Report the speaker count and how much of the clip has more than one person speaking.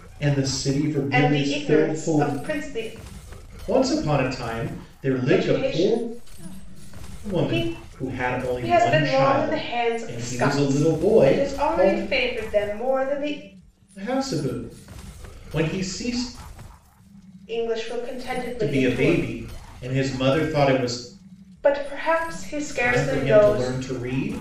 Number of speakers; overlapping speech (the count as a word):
two, about 28%